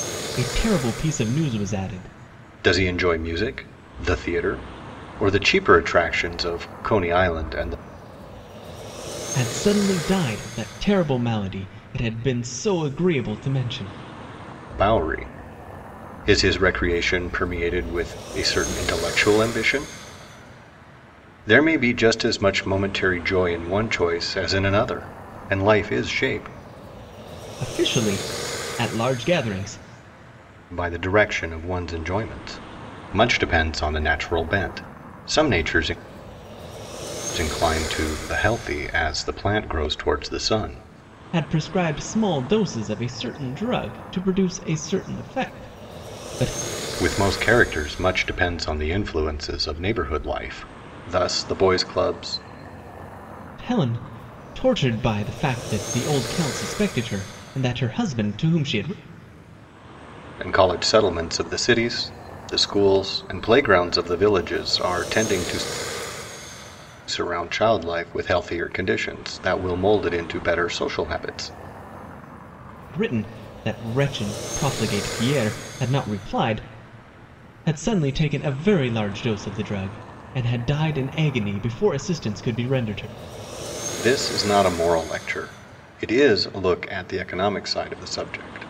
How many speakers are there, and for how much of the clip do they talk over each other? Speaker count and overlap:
2, no overlap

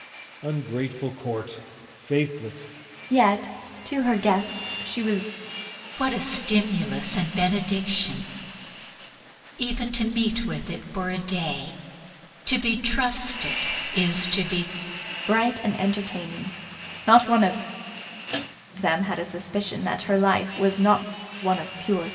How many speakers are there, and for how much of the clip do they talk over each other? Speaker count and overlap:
3, no overlap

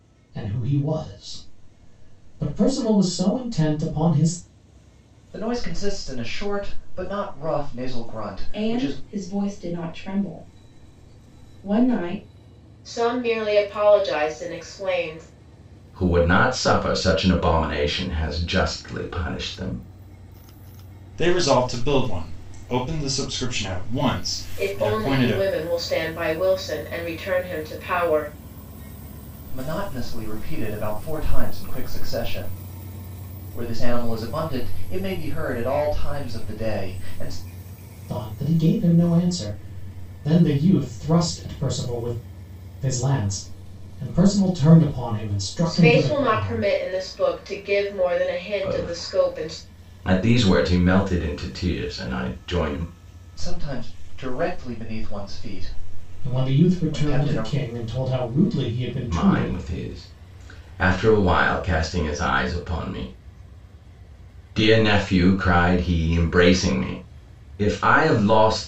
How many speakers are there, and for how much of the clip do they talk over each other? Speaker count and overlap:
6, about 8%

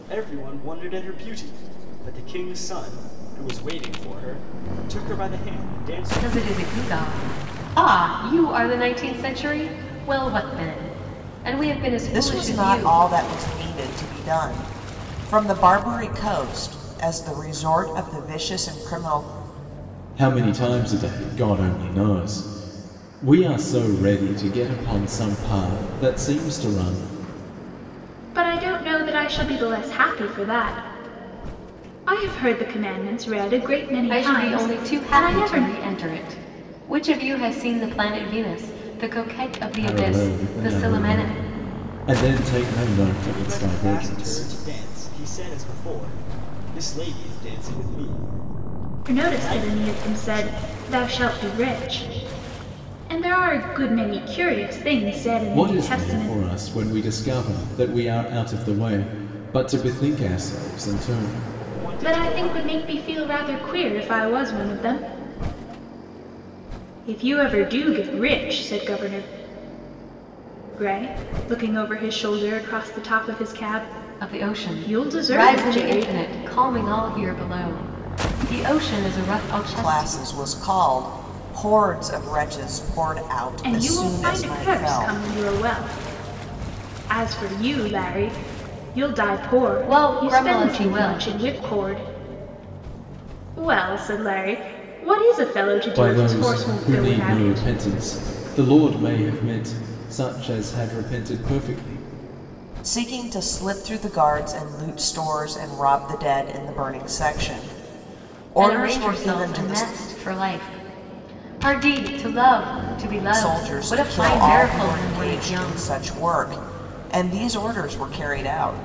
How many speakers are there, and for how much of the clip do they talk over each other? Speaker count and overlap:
5, about 18%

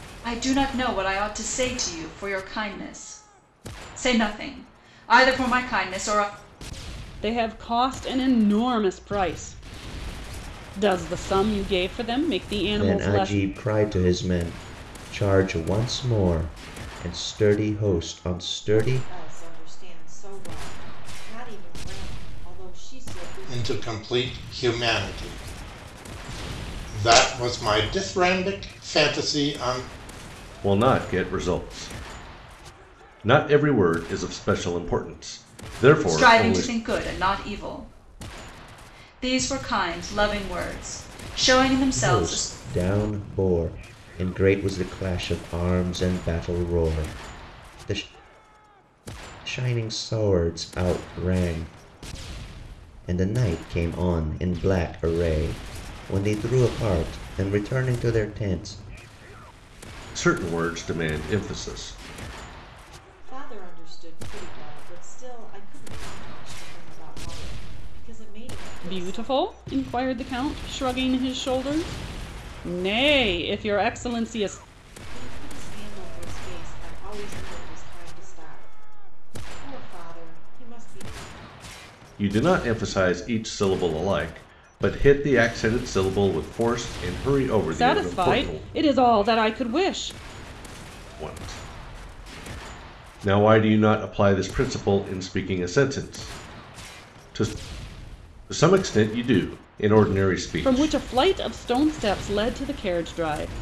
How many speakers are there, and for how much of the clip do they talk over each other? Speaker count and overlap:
6, about 4%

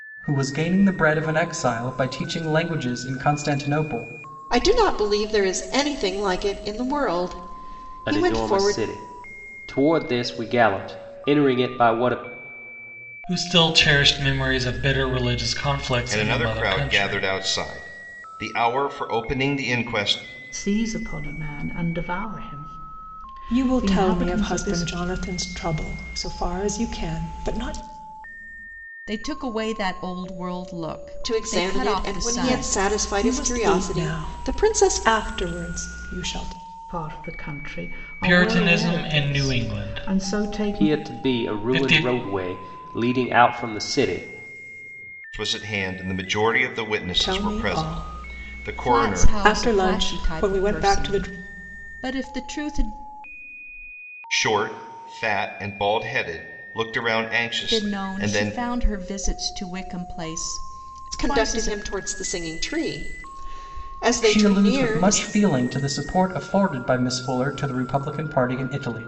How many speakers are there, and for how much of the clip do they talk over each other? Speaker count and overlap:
8, about 26%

